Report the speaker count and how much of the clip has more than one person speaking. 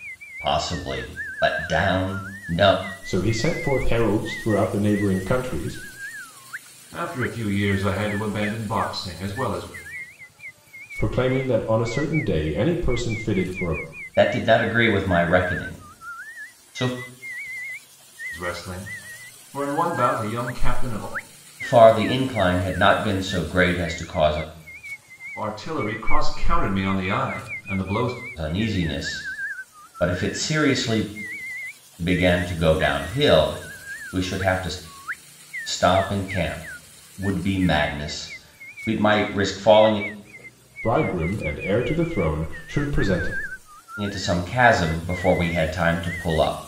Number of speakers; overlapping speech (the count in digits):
3, no overlap